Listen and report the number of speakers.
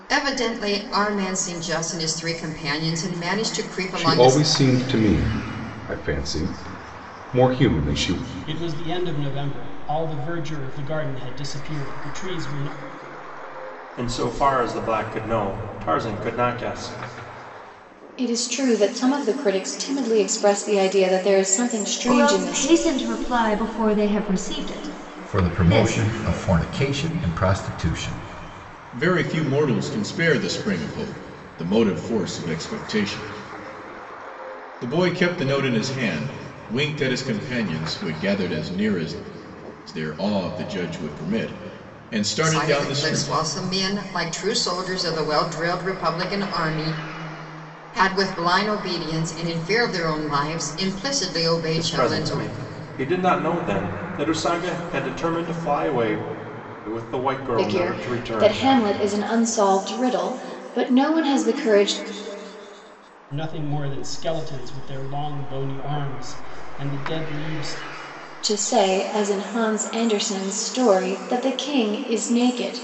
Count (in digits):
8